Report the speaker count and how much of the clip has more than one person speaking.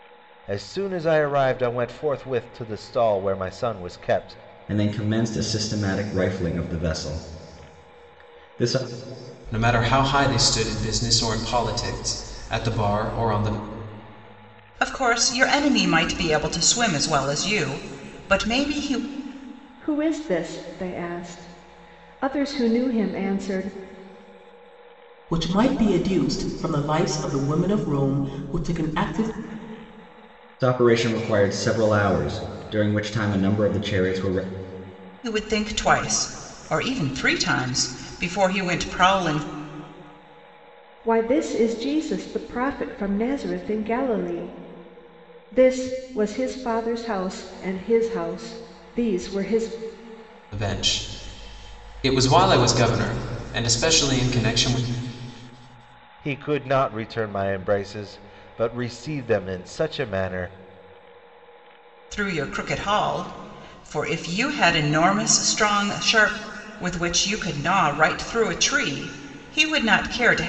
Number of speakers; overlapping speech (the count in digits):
6, no overlap